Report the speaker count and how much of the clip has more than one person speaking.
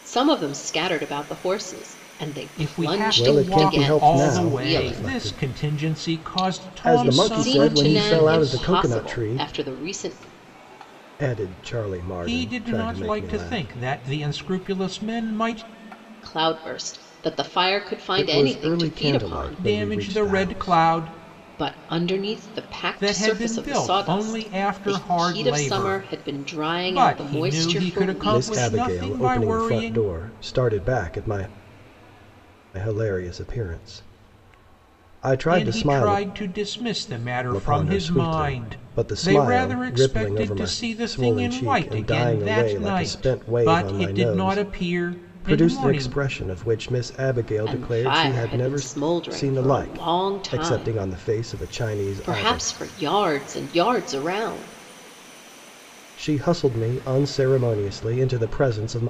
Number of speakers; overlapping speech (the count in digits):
3, about 49%